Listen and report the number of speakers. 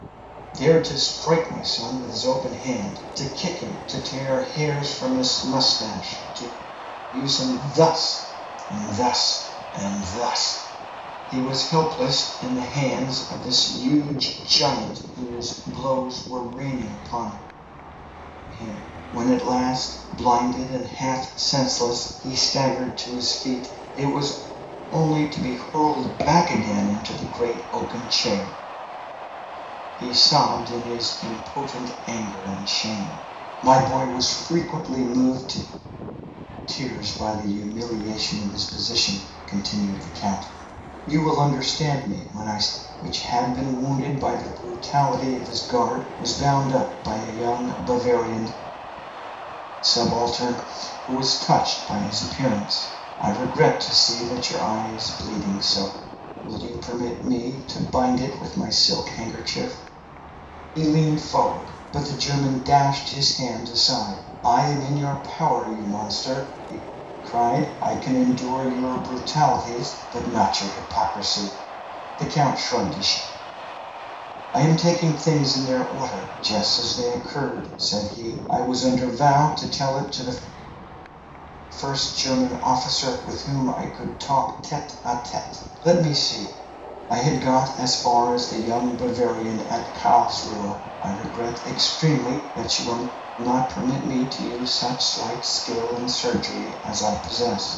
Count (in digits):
1